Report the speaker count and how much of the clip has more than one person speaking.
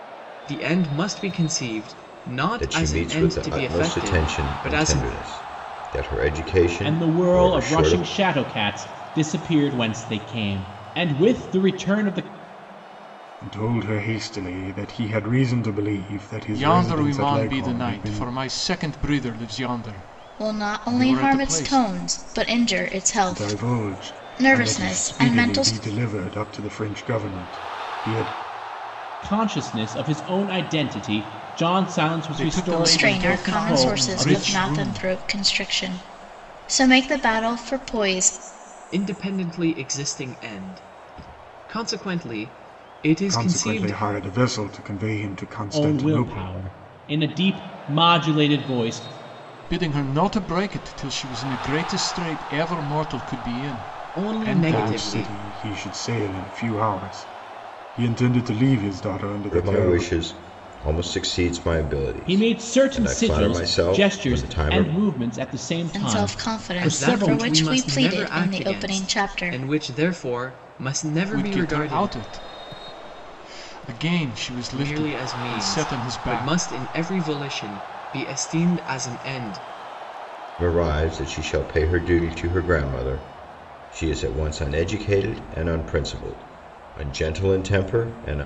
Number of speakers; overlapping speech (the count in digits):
6, about 28%